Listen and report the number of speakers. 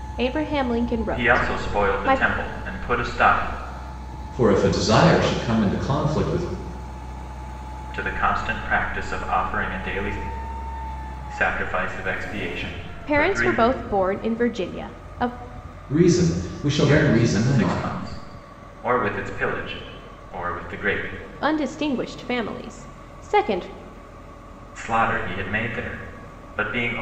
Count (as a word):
three